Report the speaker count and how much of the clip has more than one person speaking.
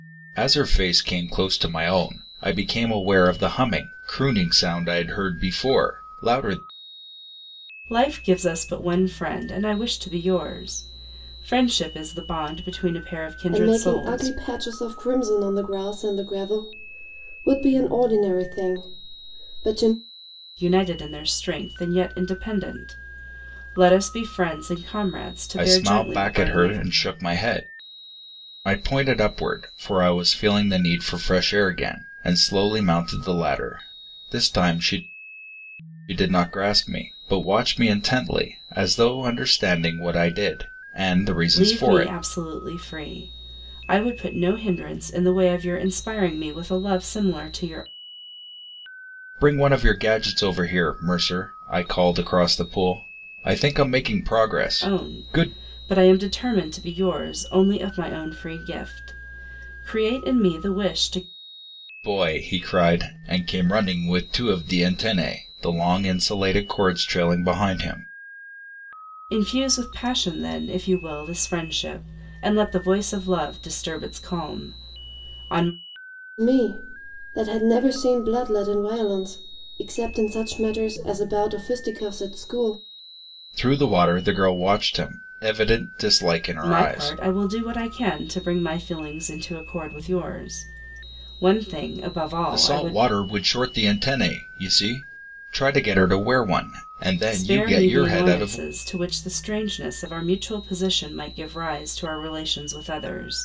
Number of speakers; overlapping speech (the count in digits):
3, about 6%